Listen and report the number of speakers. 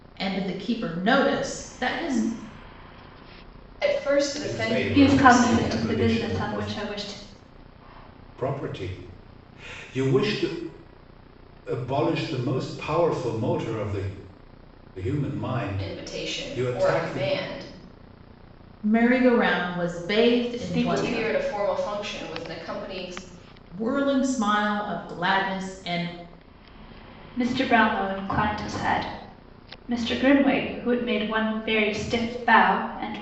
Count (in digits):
4